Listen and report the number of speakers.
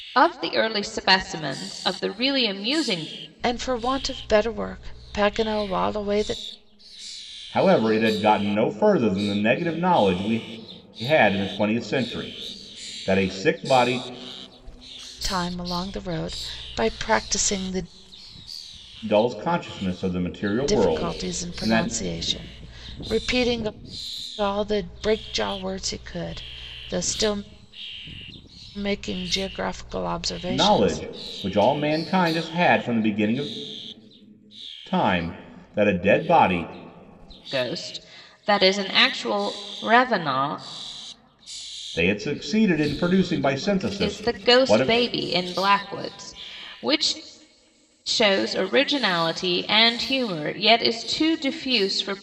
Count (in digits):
3